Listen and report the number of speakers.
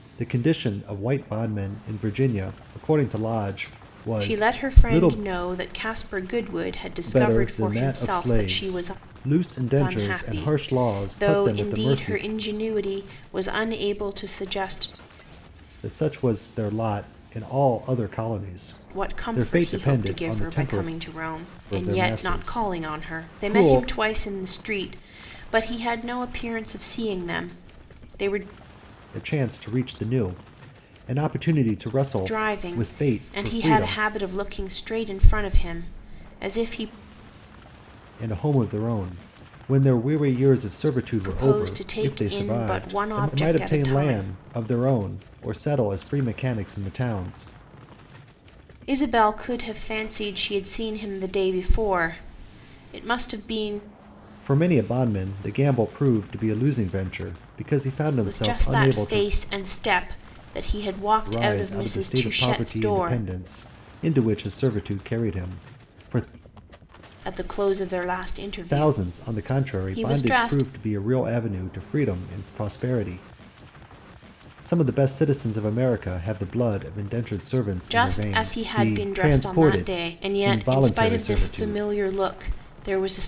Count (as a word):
two